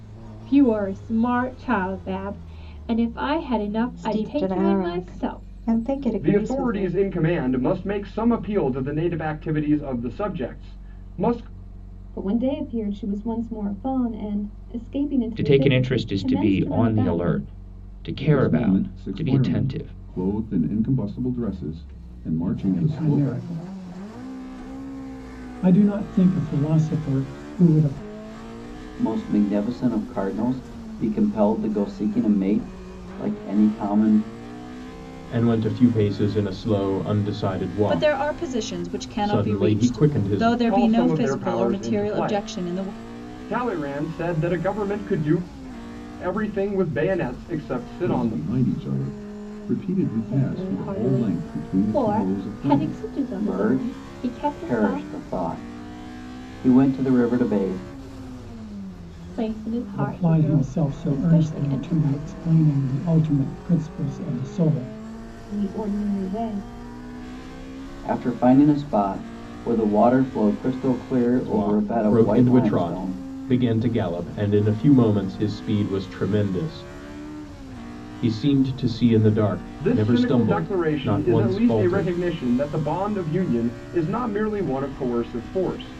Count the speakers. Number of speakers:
10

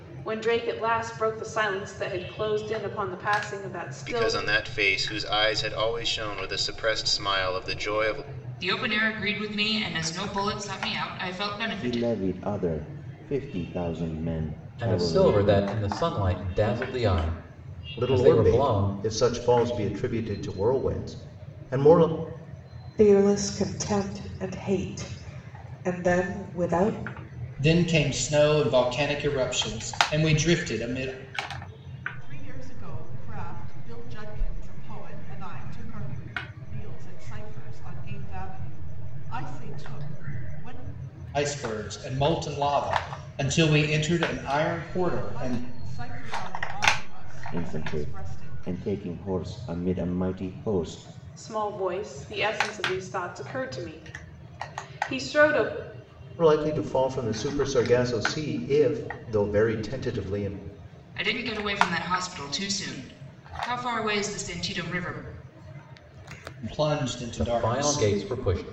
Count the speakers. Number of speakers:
9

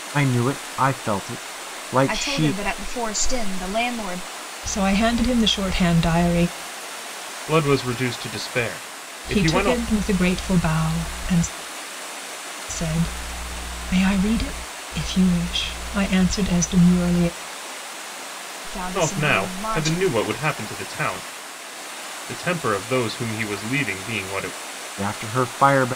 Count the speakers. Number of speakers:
4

